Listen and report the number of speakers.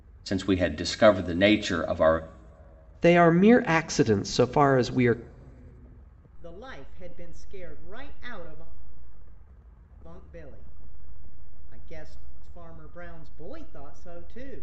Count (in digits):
3